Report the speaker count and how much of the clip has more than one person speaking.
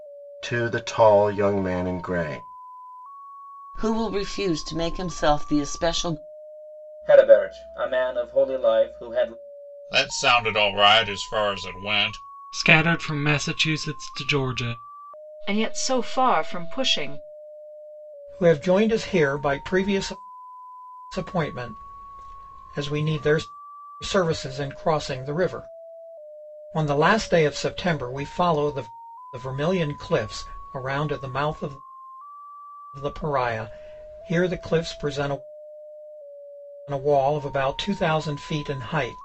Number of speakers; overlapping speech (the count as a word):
seven, no overlap